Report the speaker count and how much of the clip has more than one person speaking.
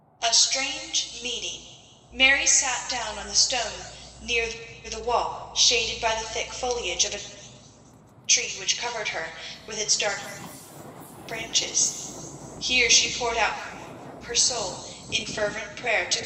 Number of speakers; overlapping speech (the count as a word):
one, no overlap